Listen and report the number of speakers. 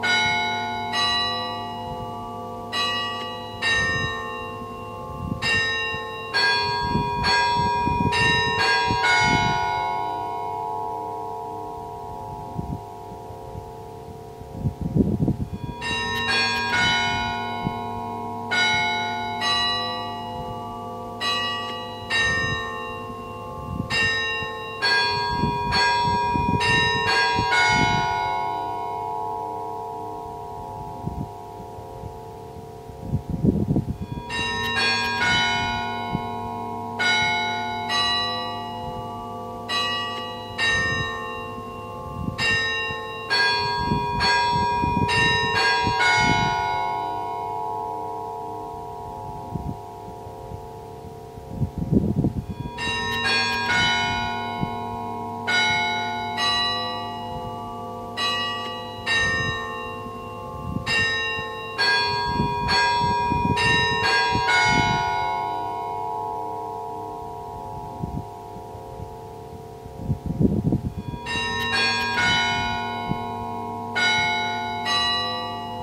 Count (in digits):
0